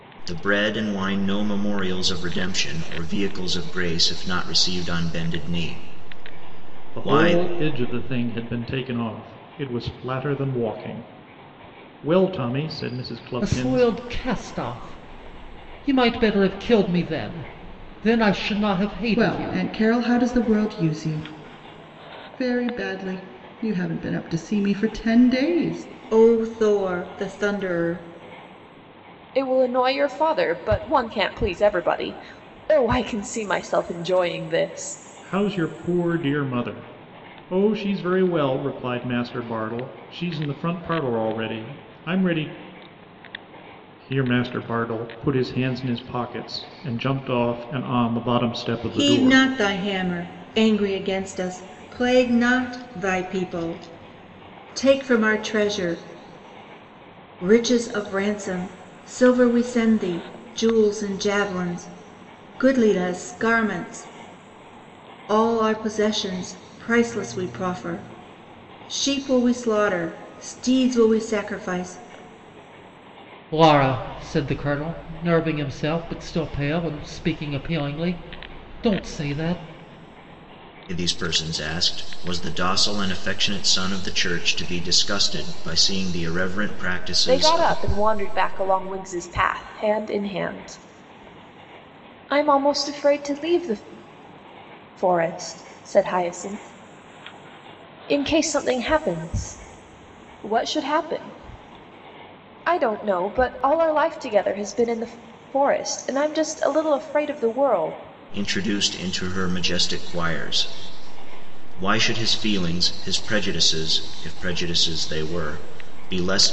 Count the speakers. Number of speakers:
six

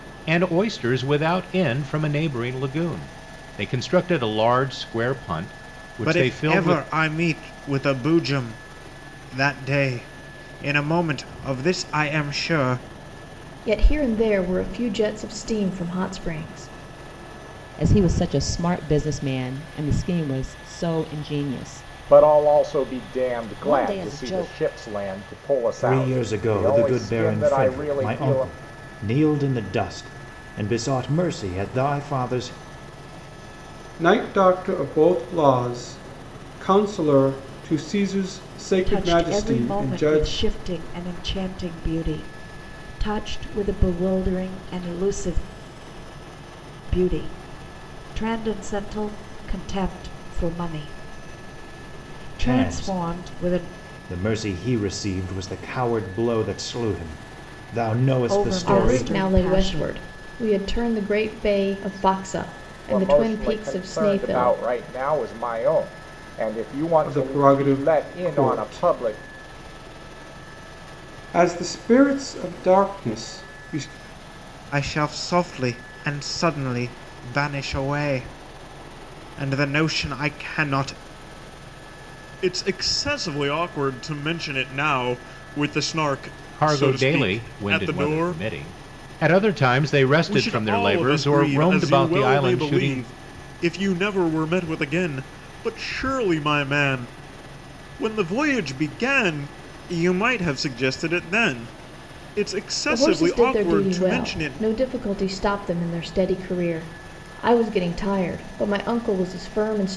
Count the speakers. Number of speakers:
eight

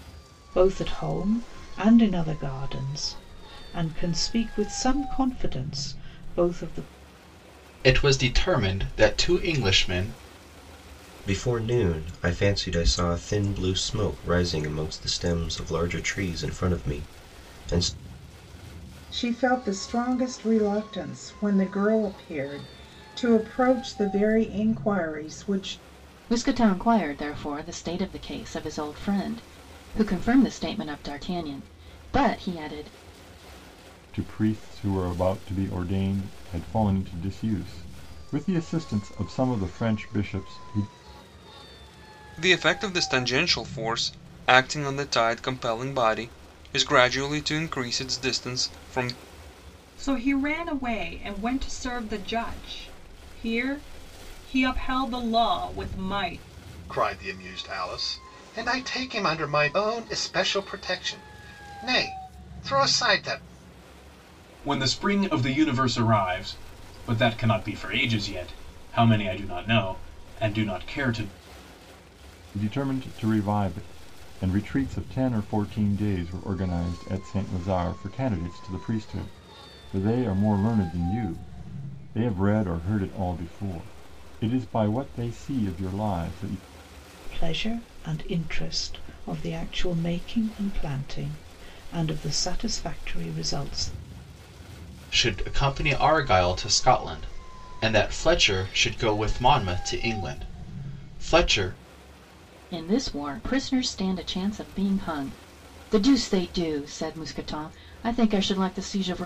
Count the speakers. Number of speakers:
ten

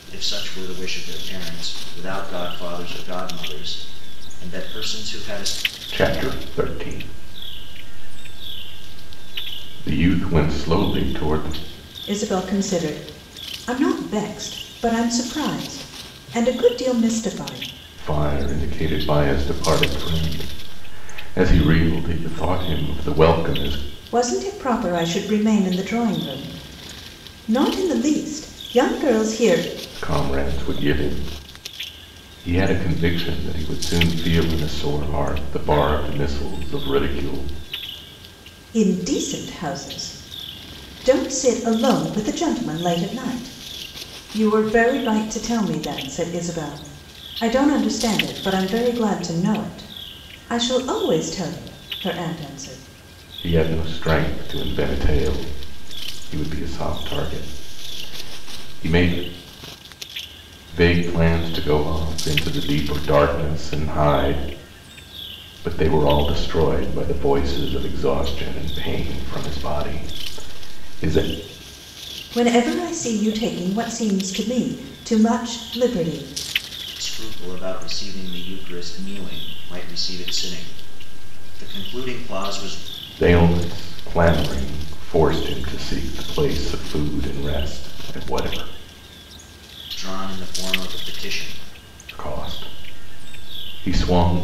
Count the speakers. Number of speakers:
three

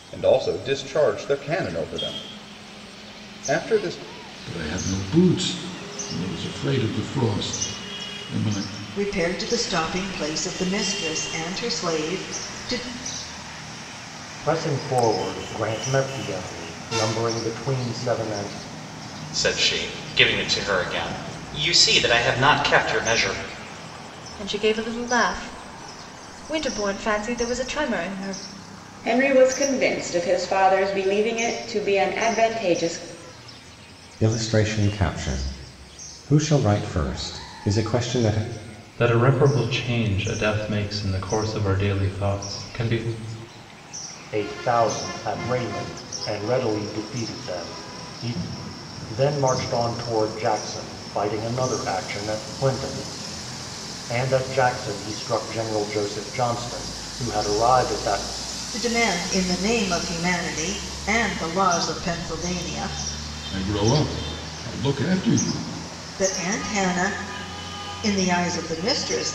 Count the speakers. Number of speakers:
nine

